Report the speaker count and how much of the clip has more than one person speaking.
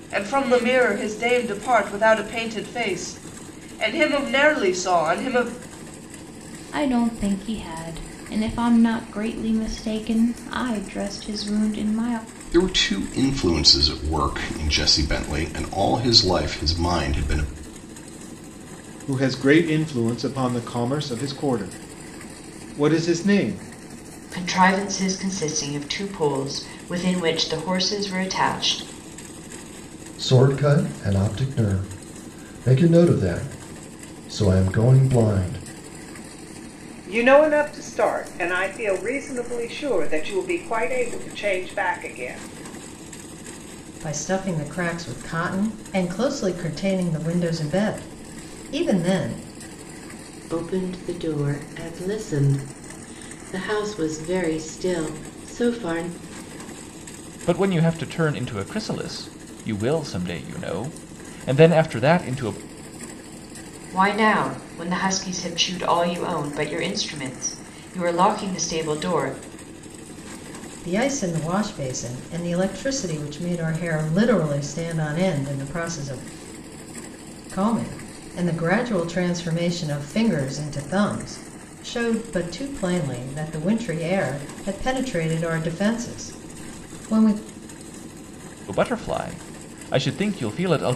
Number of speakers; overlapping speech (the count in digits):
10, no overlap